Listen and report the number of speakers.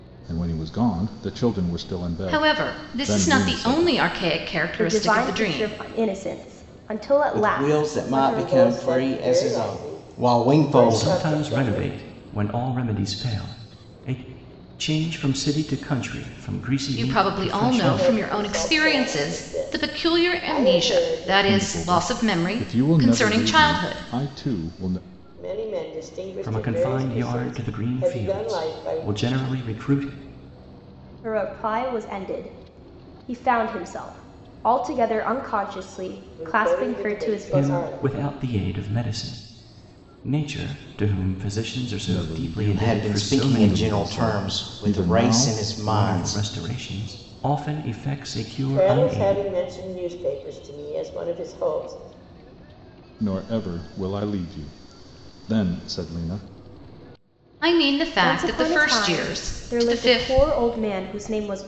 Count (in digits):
6